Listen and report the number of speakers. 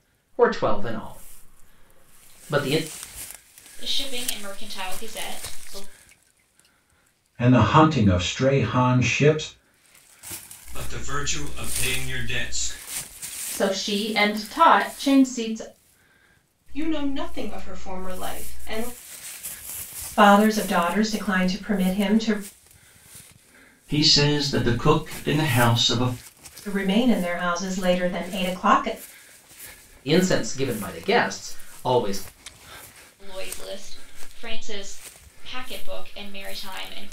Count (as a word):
eight